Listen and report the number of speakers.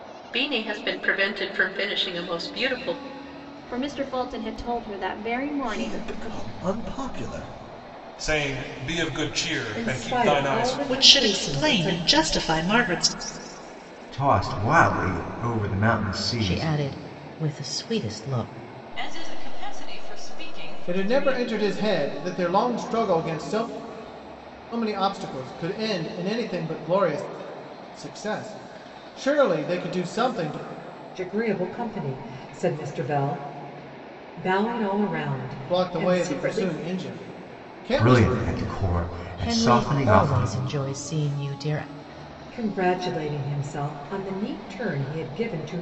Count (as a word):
ten